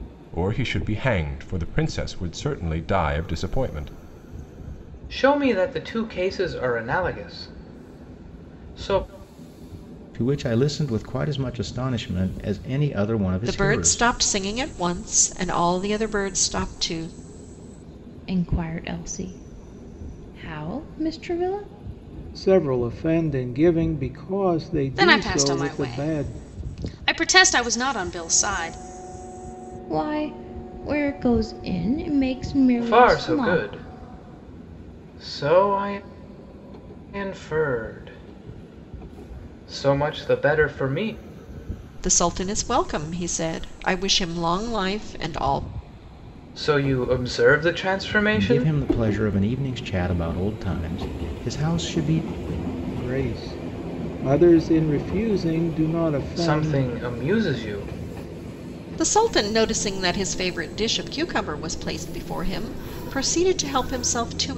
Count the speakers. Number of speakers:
7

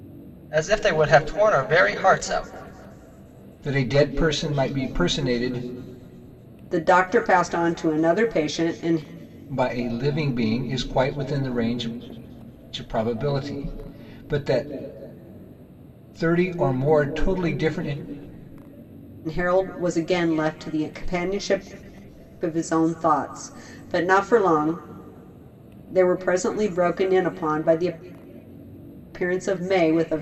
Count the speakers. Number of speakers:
3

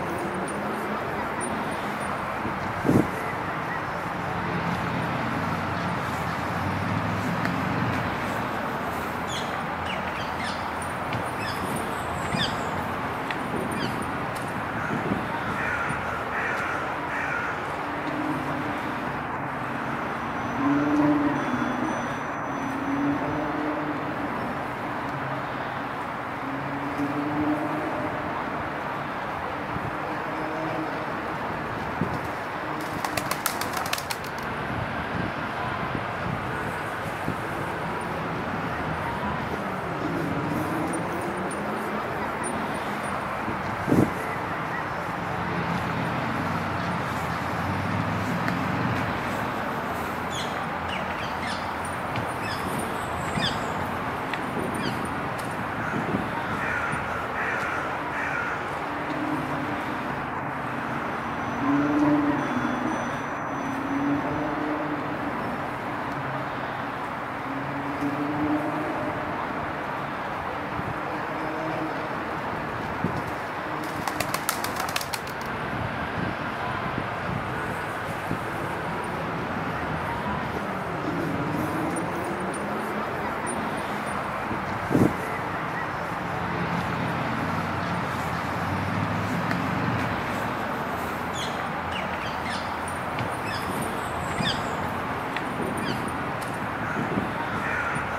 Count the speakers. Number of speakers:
0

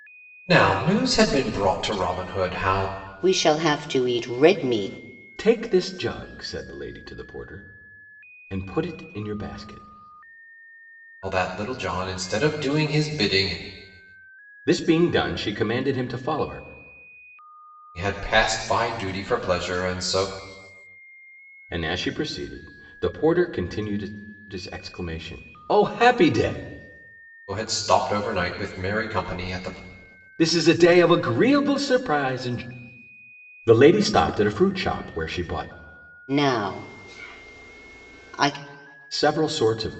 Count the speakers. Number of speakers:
3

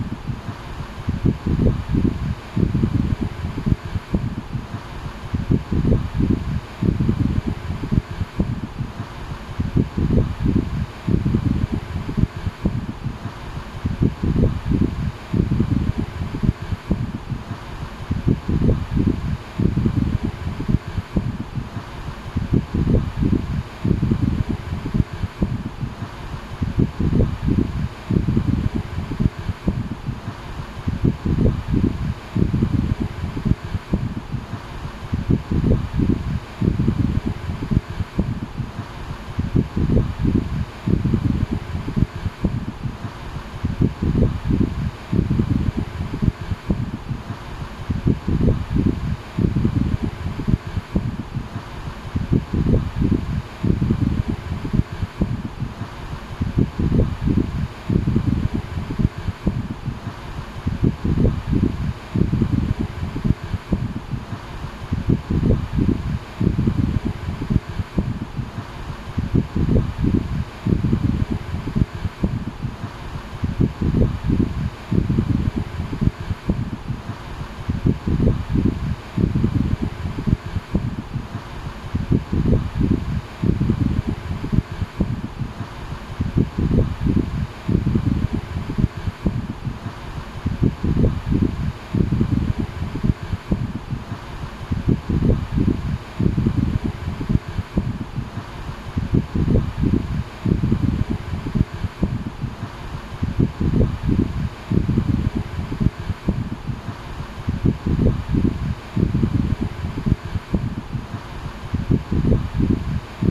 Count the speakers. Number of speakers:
0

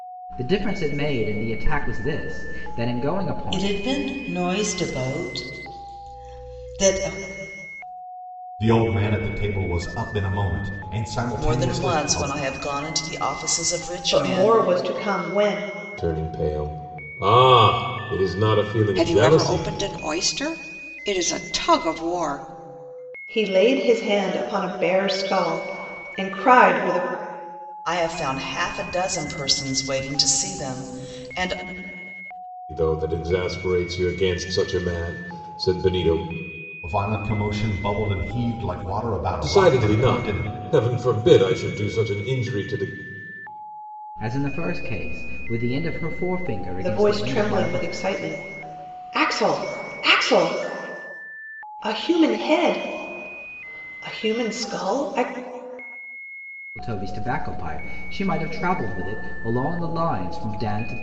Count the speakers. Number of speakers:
7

